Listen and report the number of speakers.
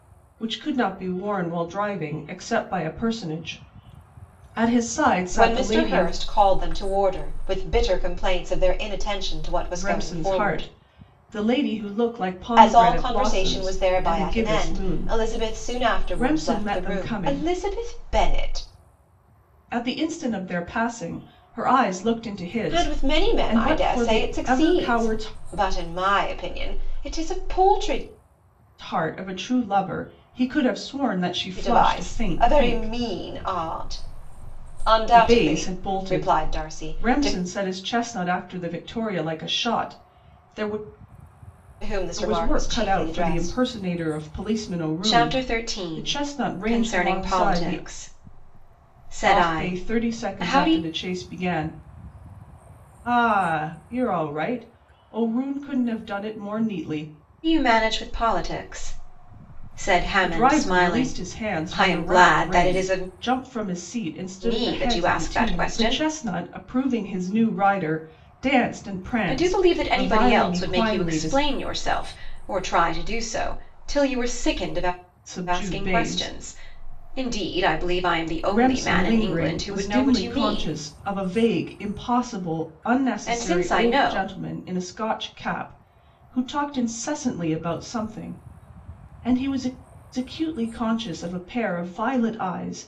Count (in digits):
2